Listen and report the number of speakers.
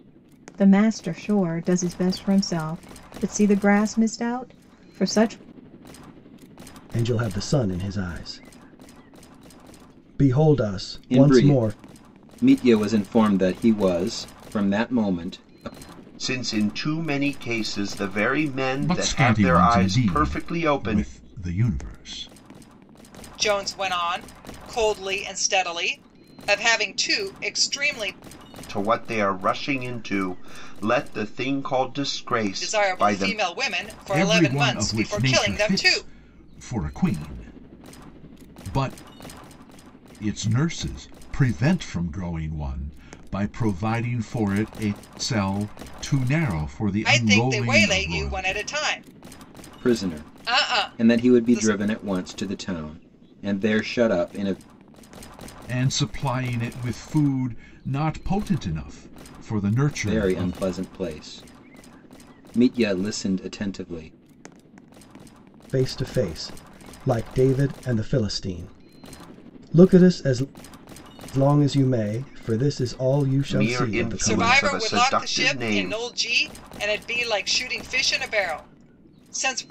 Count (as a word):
six